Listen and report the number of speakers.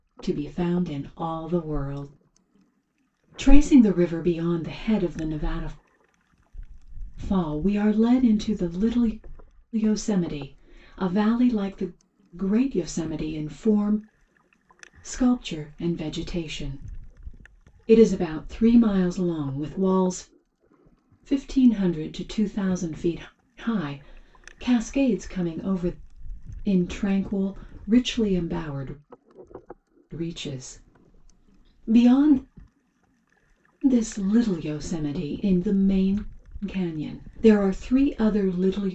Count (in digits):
1